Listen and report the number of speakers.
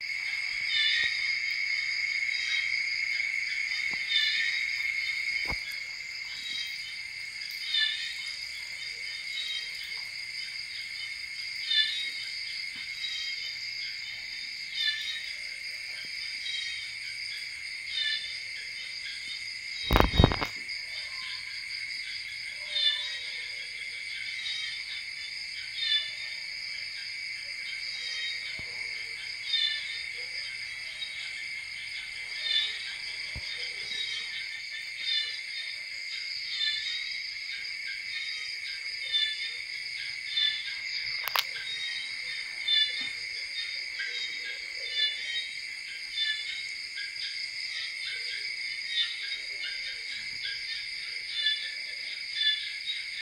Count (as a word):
zero